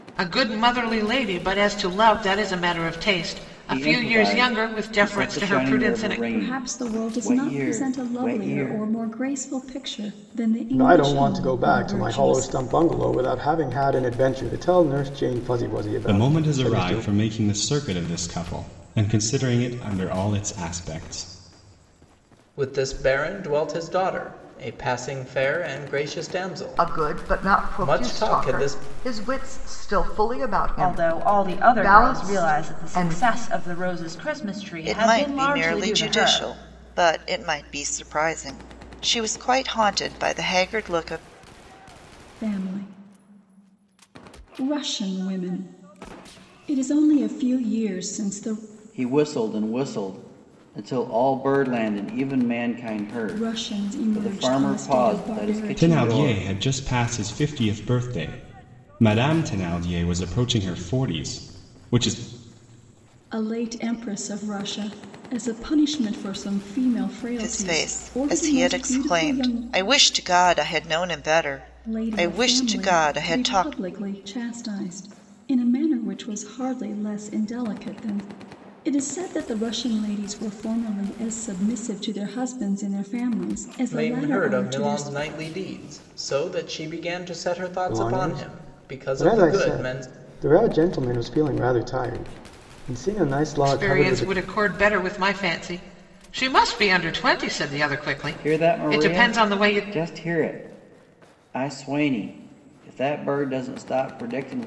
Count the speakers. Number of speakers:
9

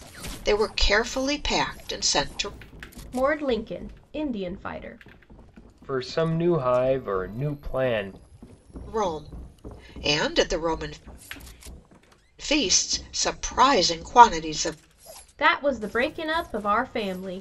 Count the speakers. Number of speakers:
3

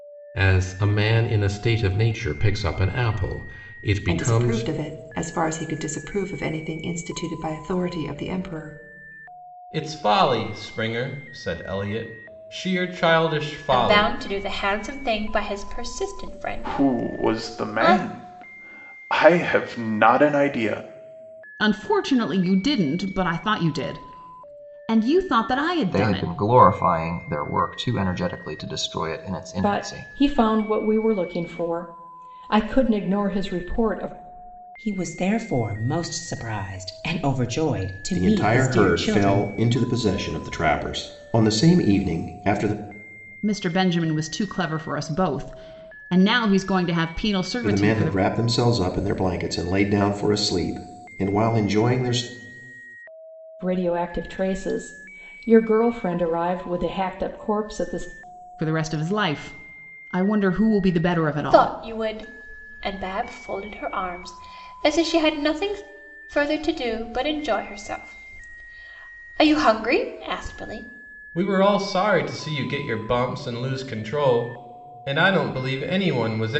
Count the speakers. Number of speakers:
10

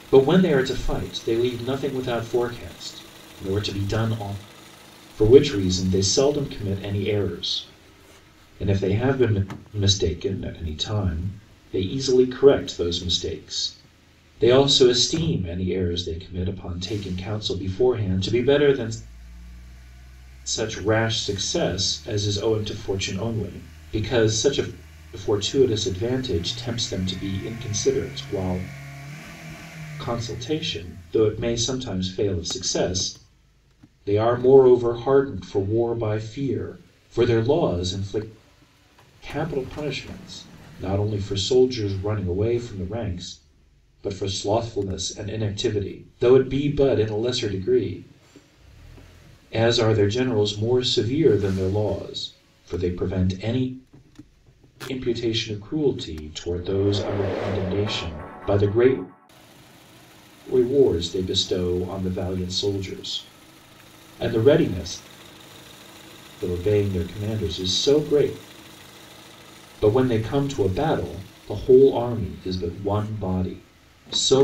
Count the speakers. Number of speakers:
1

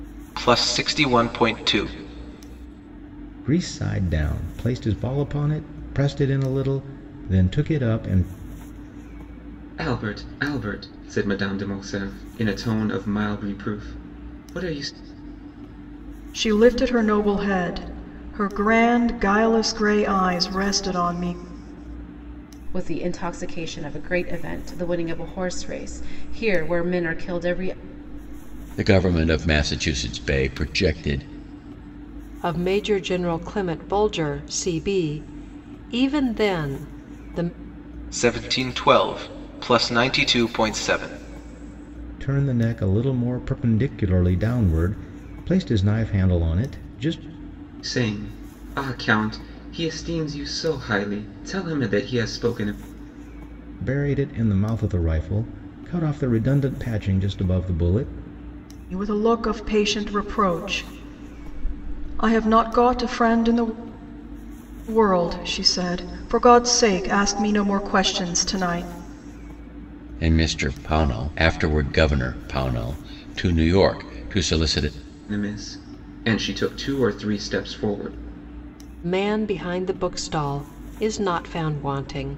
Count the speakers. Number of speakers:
7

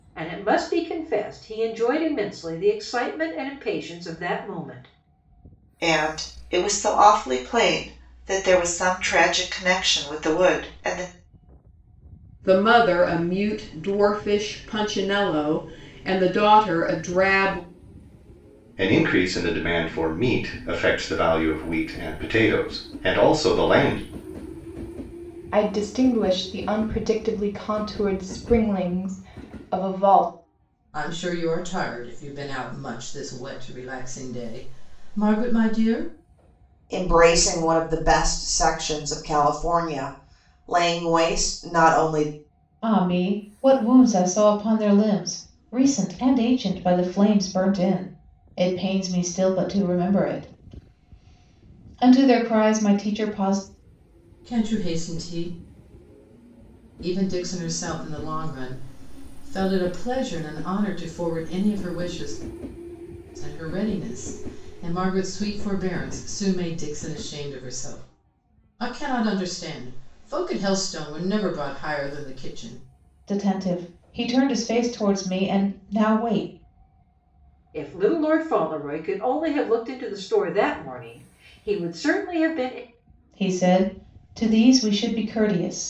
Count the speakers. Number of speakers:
8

